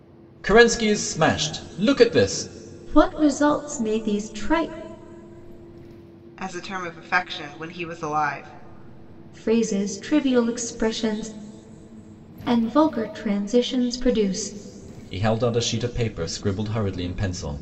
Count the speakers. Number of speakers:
three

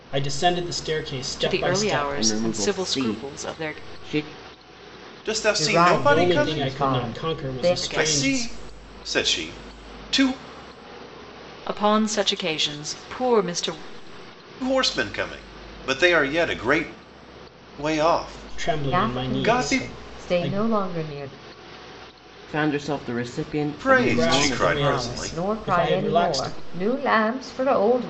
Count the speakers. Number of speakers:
five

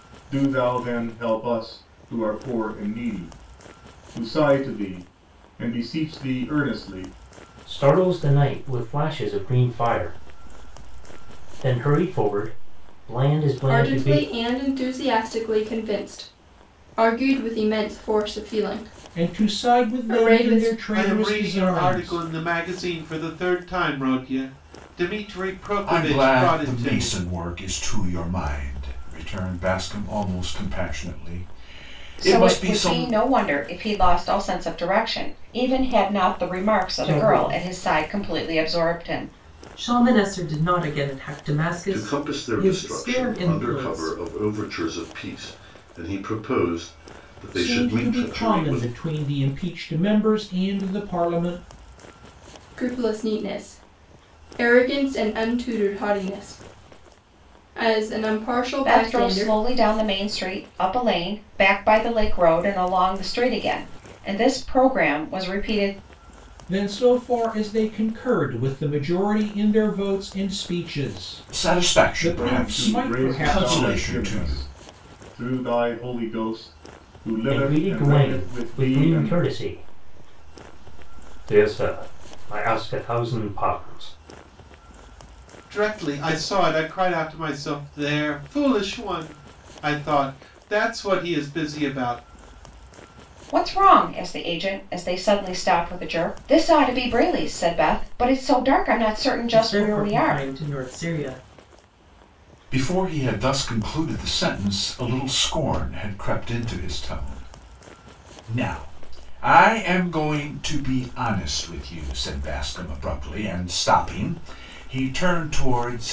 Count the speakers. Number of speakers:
nine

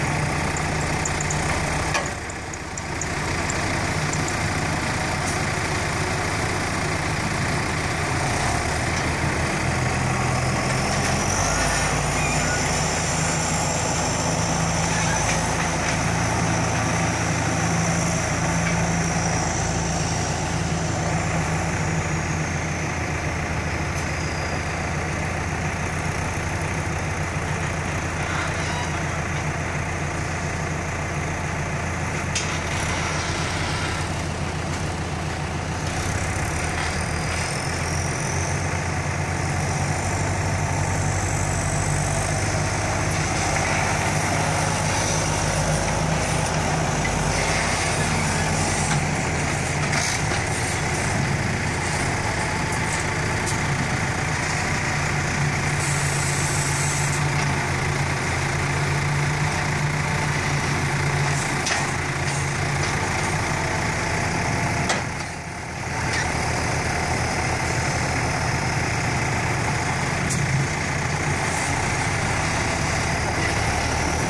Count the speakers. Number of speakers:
zero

